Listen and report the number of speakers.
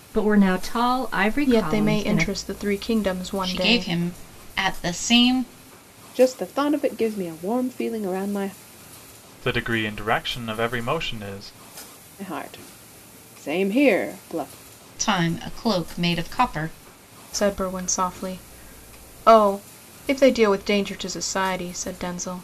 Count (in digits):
5